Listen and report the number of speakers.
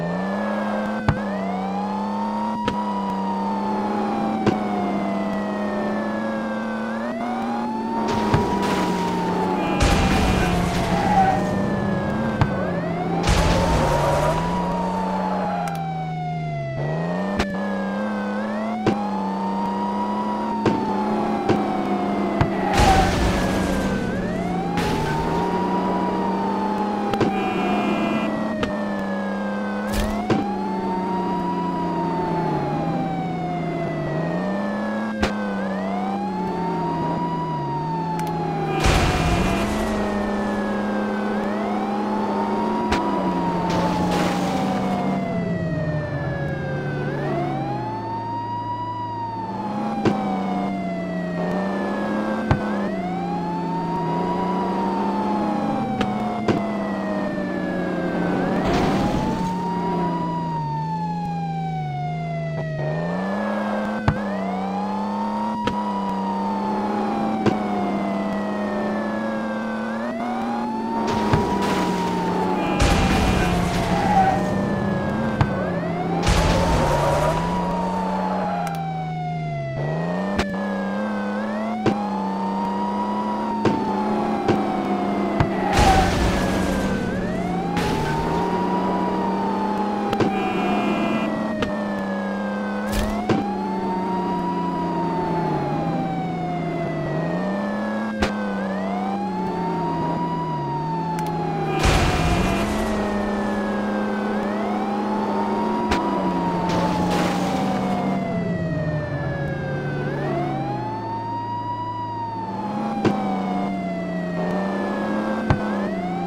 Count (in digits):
0